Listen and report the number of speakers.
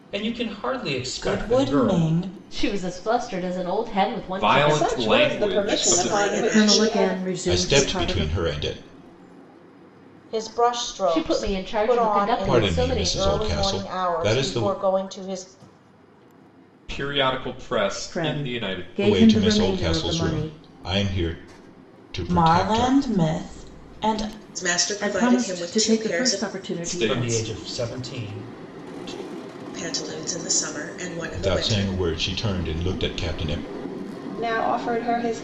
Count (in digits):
9